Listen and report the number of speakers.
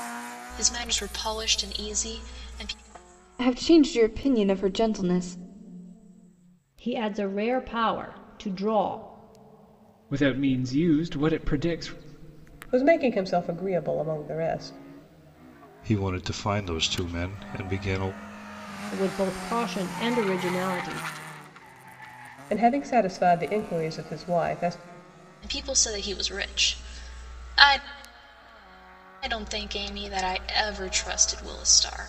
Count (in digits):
6